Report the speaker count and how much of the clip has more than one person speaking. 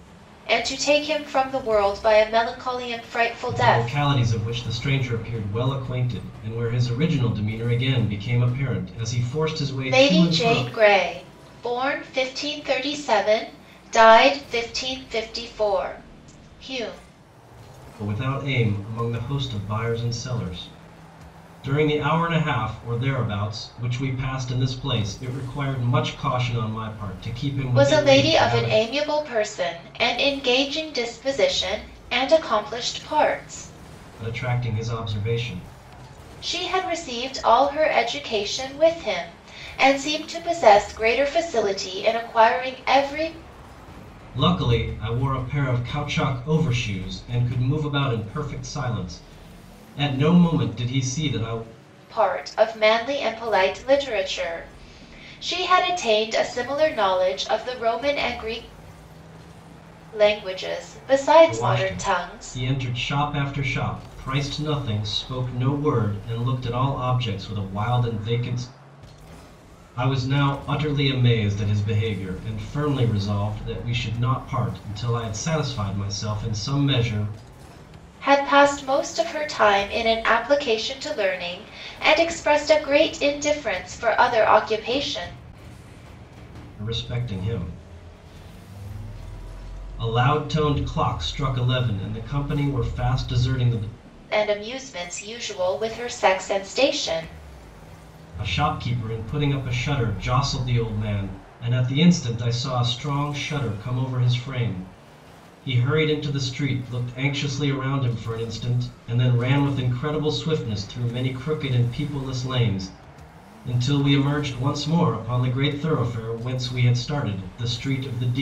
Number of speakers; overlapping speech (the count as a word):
two, about 3%